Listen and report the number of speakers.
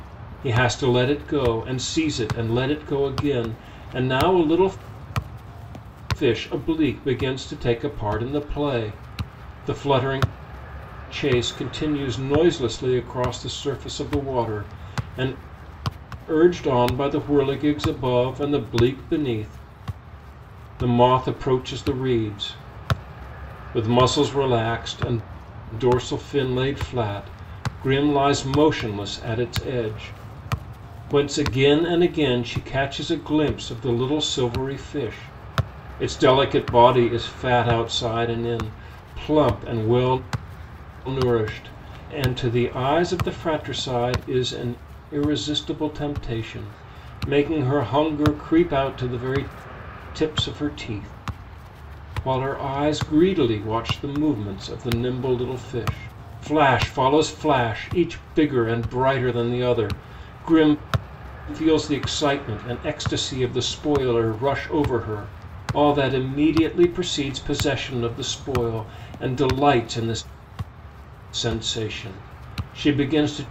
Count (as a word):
one